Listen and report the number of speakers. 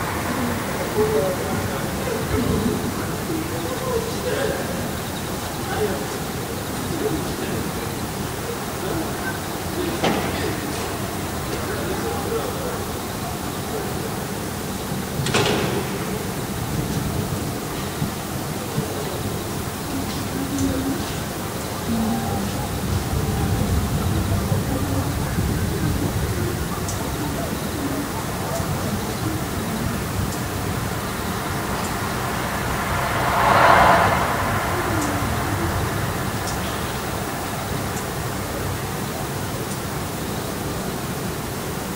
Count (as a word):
zero